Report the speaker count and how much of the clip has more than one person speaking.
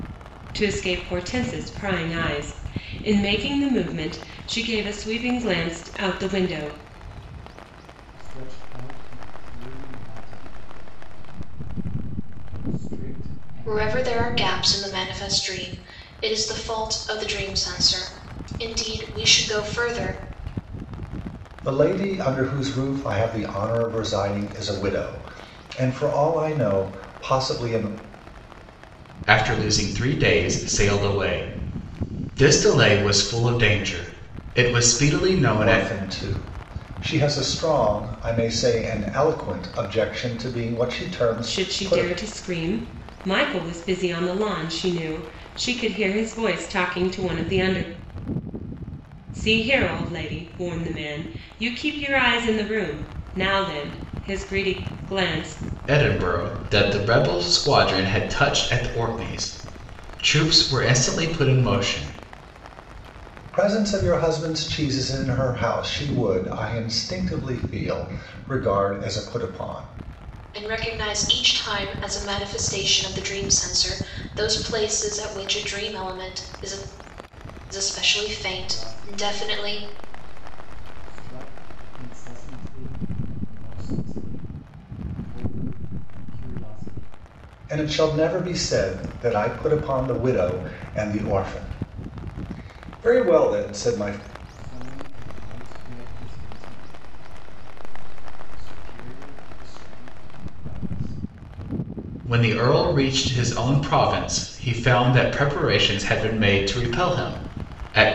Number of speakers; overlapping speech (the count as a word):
five, about 3%